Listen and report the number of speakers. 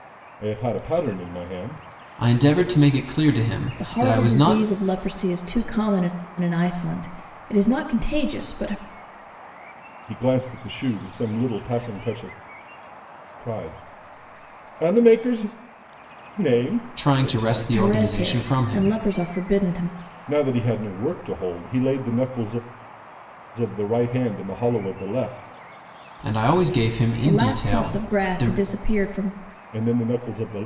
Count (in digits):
3